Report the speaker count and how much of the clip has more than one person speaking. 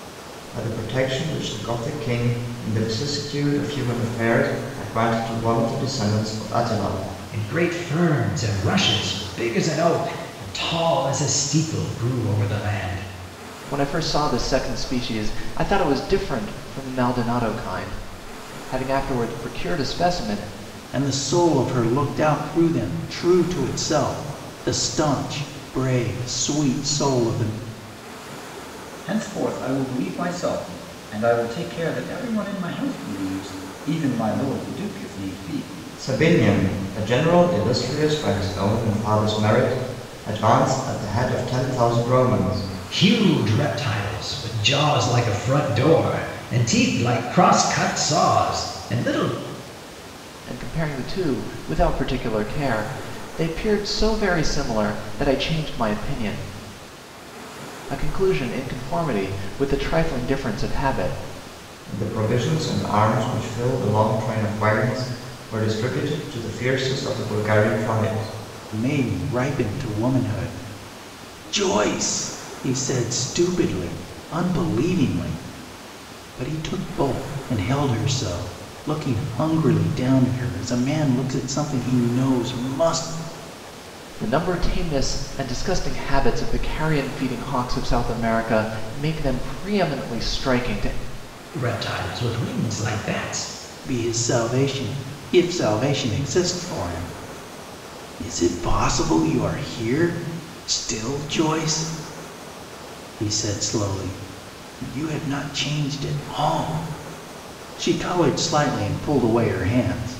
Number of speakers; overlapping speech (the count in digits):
5, no overlap